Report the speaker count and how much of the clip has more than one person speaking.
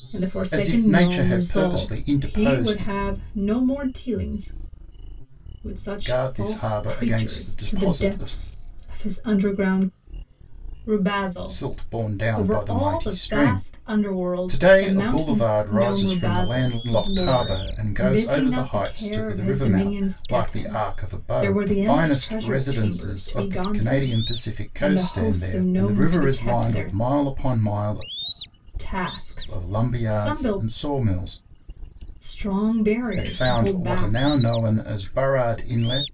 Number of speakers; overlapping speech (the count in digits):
2, about 58%